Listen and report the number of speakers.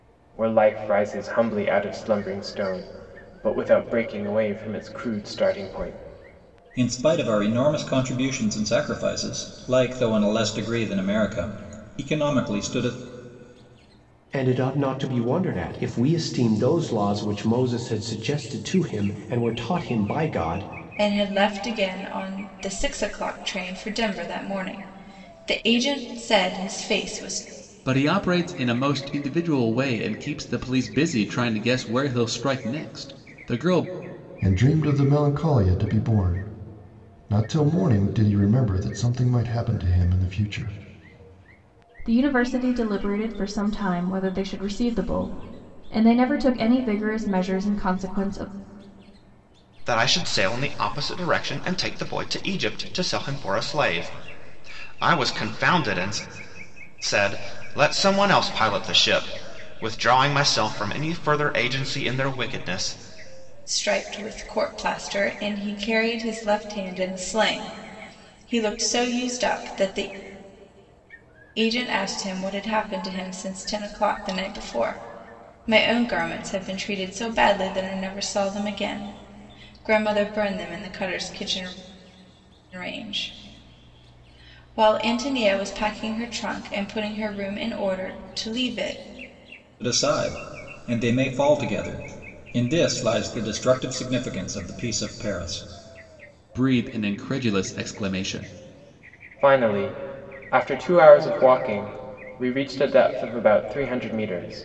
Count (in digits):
8